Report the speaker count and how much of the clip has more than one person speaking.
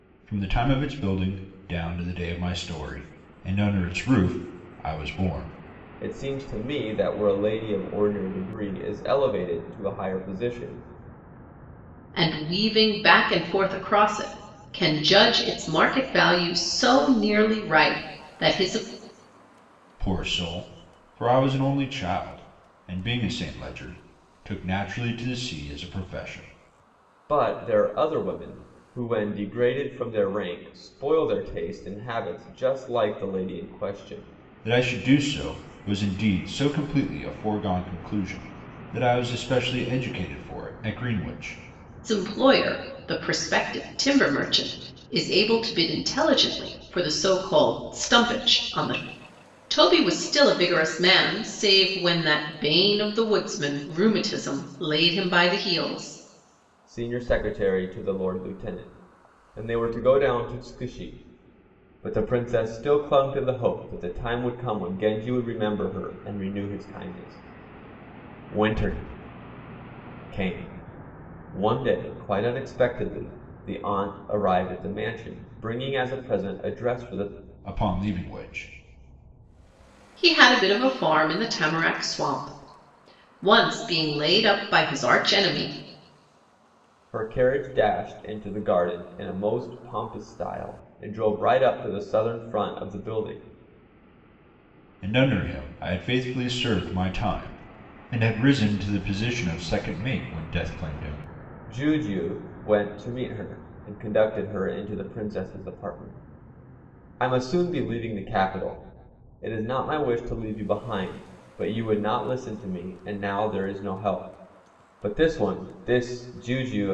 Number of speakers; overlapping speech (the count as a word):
three, no overlap